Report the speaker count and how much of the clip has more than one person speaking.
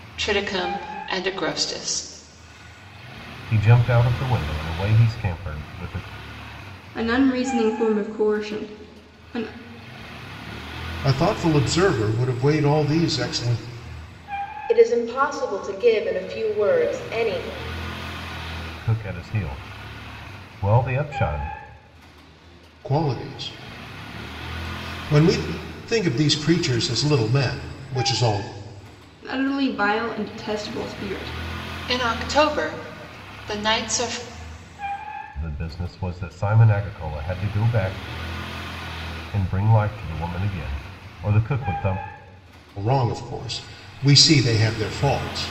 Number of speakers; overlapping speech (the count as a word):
five, no overlap